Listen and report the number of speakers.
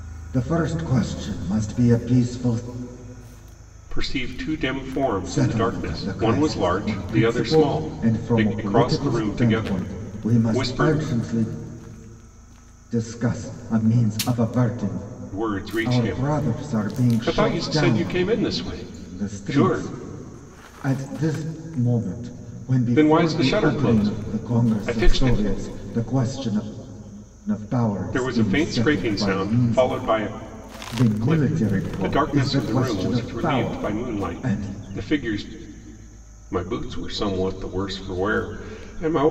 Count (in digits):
2